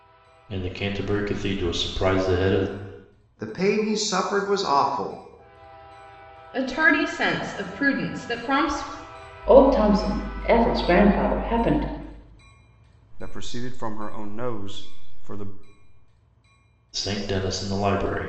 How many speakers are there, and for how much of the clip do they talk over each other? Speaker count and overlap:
five, no overlap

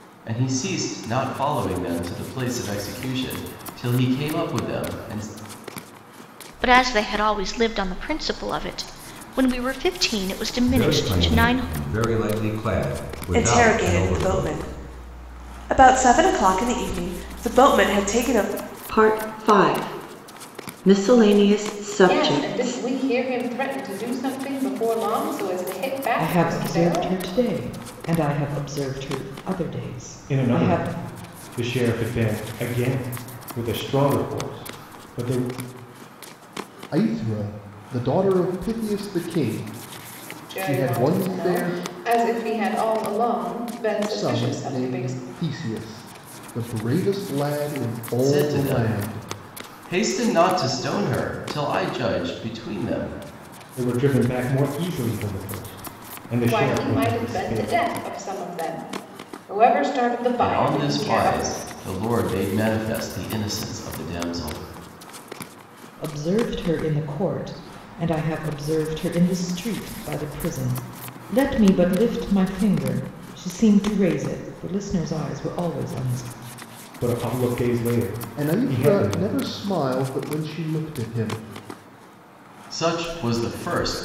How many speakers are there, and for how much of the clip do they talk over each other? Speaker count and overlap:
nine, about 14%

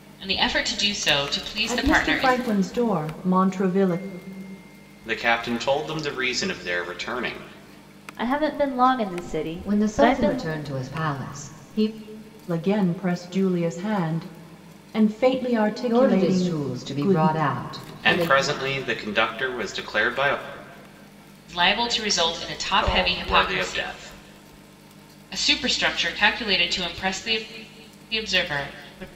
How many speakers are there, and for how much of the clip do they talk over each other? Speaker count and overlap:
five, about 15%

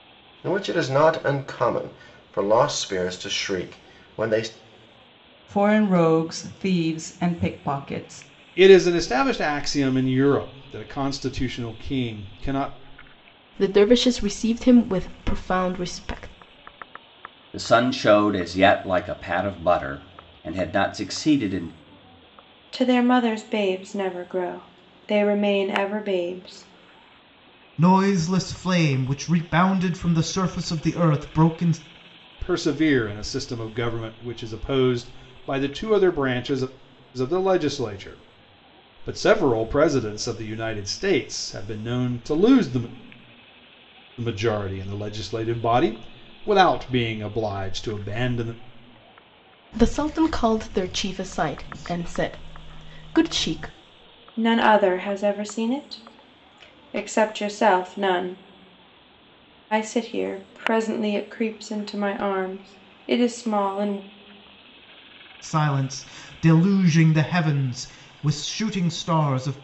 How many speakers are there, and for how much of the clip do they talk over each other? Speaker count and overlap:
seven, no overlap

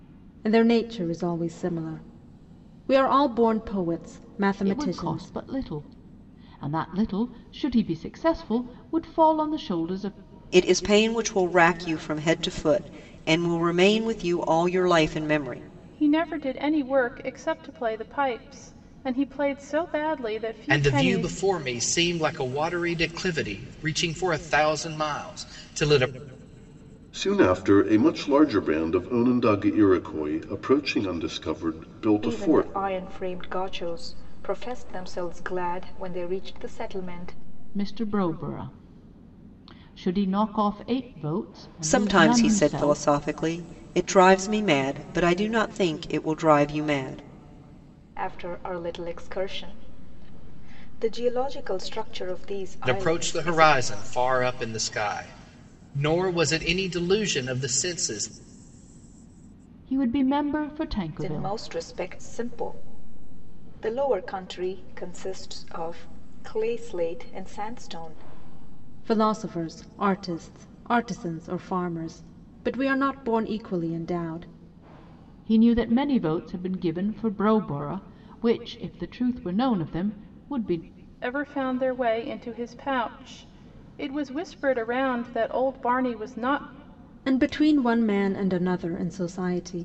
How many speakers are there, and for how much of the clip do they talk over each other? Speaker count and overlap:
seven, about 5%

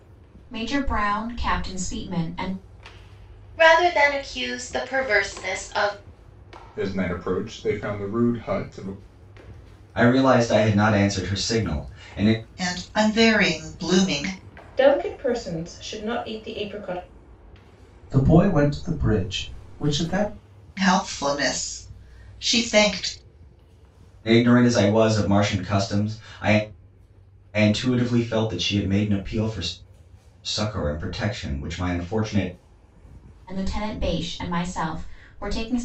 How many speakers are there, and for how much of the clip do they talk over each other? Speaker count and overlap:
seven, no overlap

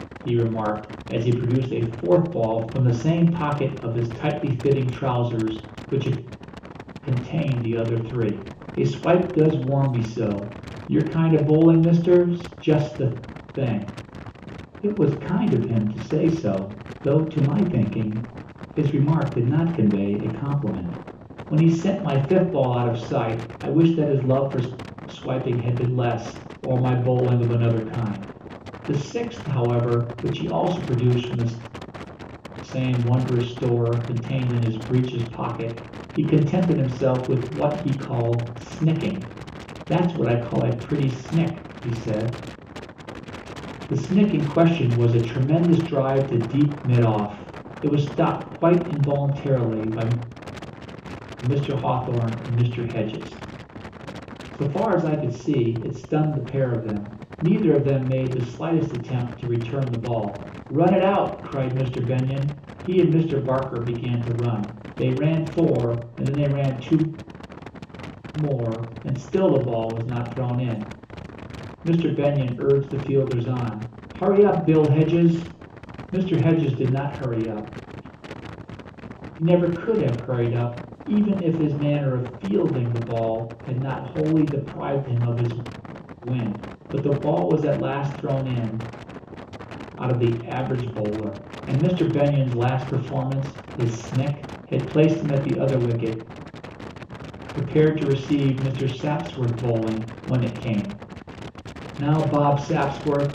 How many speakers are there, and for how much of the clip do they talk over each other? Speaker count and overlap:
one, no overlap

